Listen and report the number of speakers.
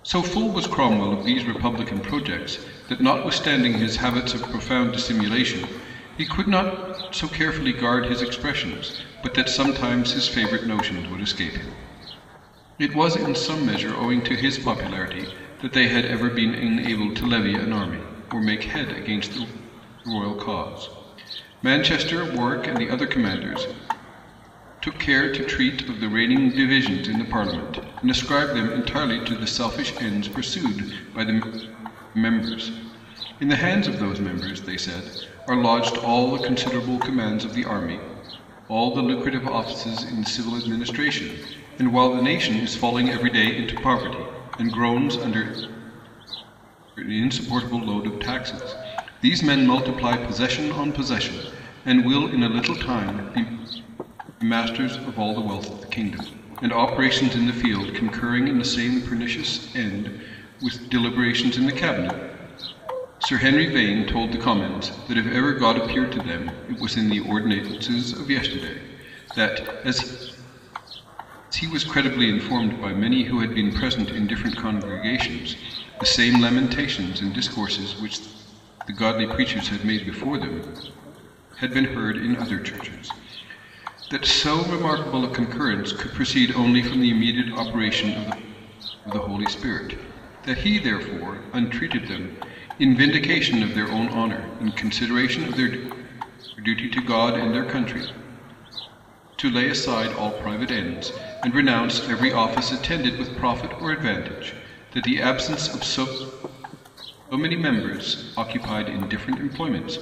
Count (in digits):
1